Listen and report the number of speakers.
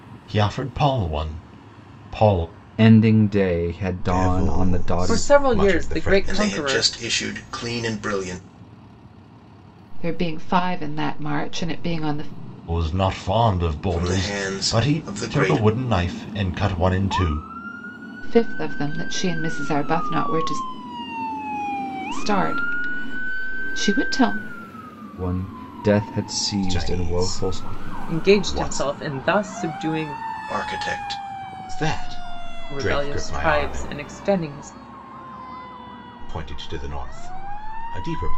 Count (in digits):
6